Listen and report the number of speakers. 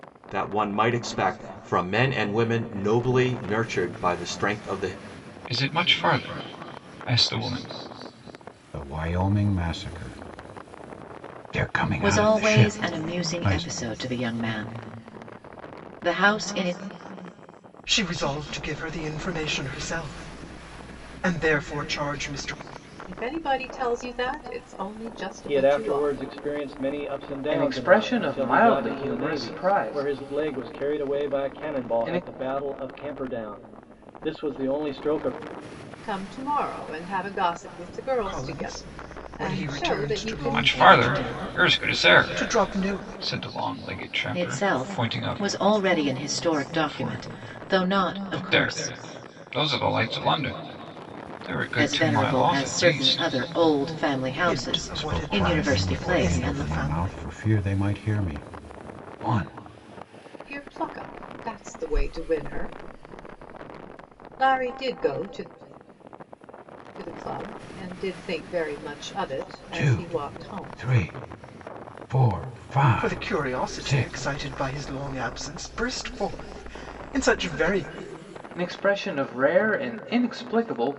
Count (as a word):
eight